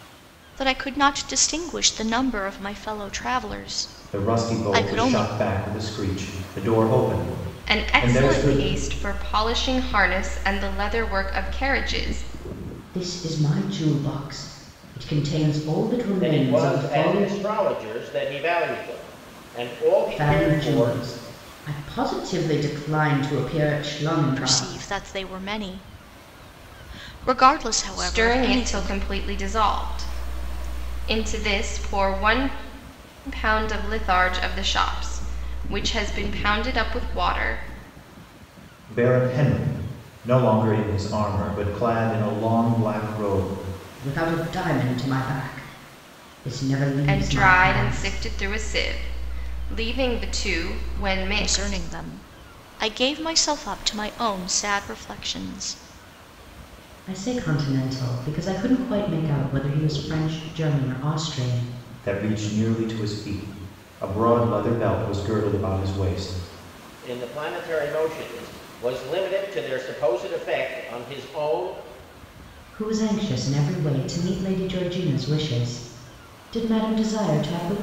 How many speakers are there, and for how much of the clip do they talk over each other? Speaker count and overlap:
5, about 10%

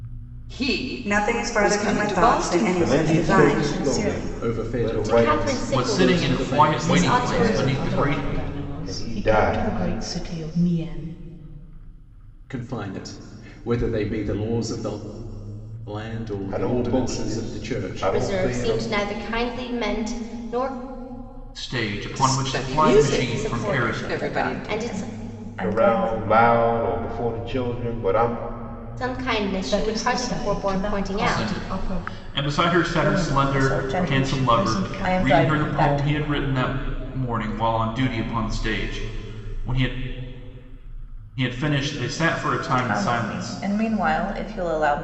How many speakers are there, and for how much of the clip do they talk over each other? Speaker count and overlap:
8, about 47%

